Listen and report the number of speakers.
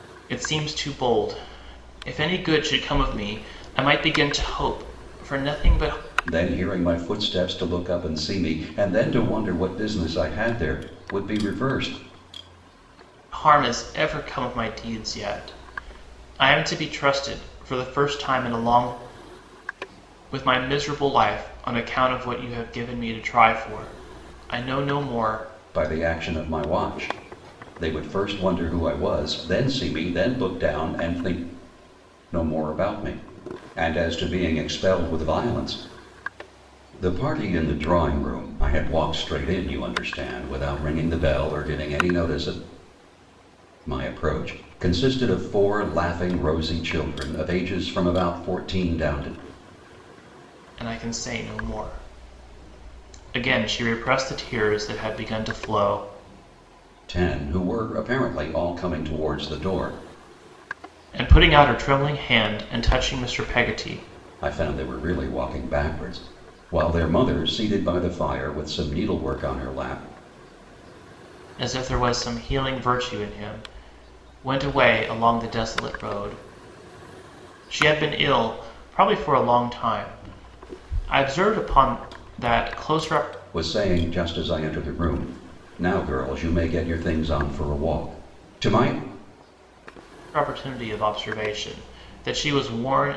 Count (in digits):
2